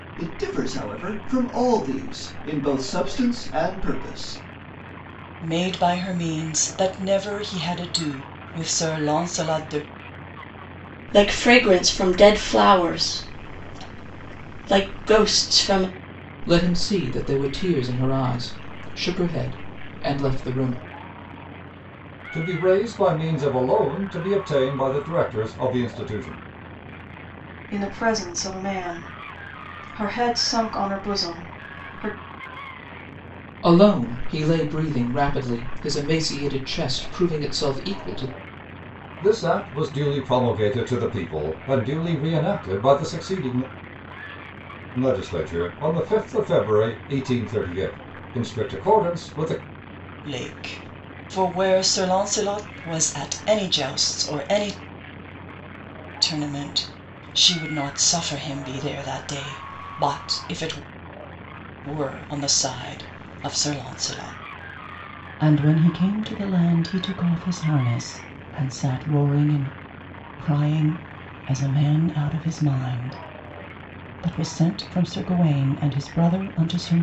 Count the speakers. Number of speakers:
six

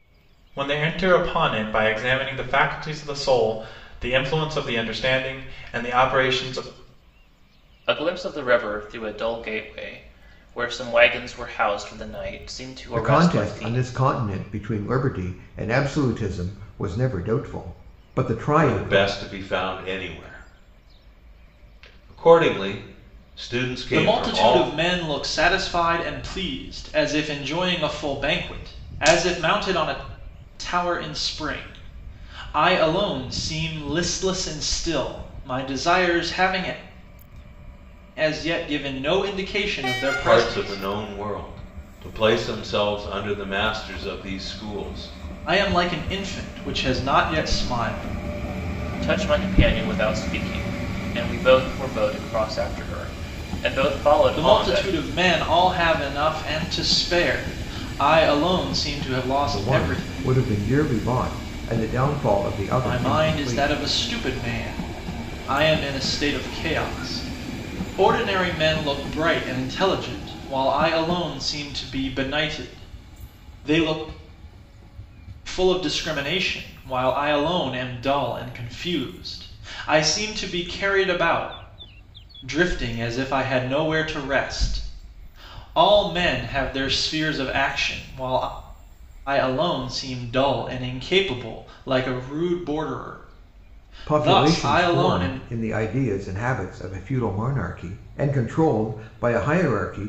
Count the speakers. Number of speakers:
five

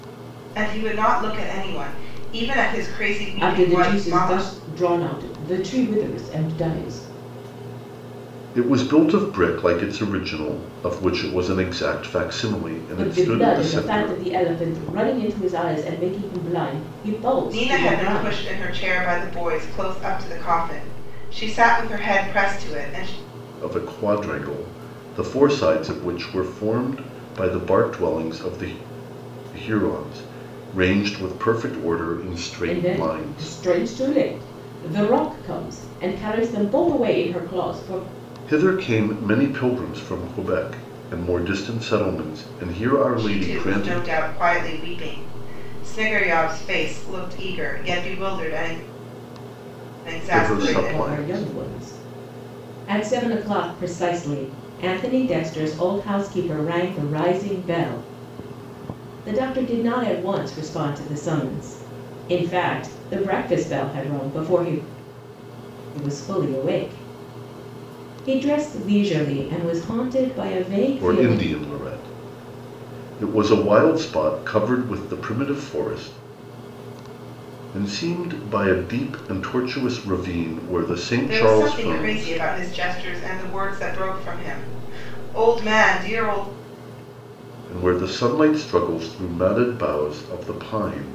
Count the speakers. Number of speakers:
three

